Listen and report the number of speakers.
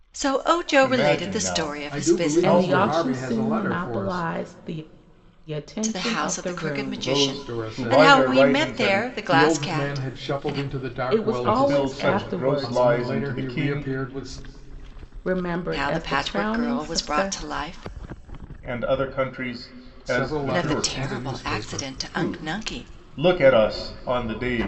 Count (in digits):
4